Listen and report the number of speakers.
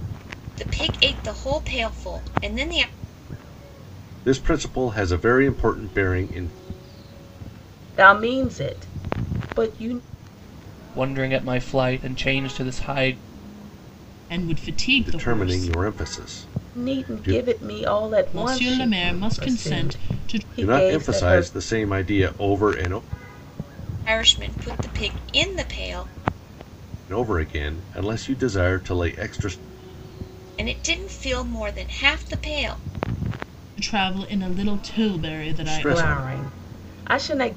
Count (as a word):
five